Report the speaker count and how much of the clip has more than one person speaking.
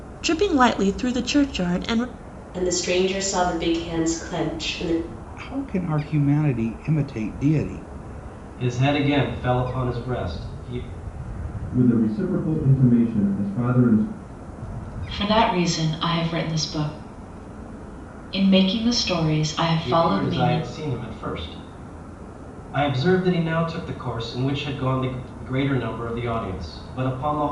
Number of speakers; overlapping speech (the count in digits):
6, about 3%